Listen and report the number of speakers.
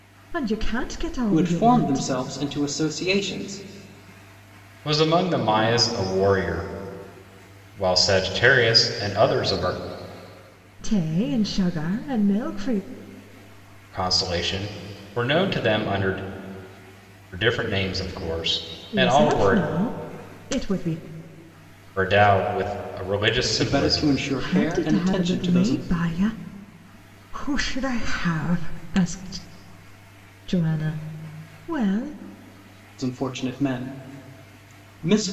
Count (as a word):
three